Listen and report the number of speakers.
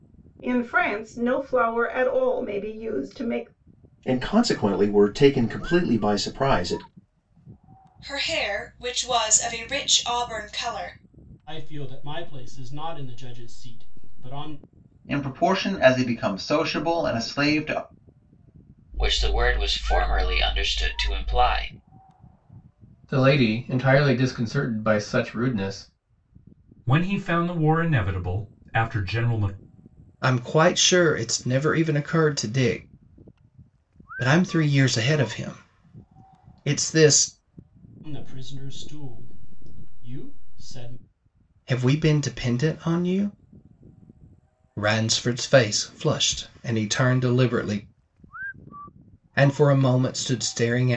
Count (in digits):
9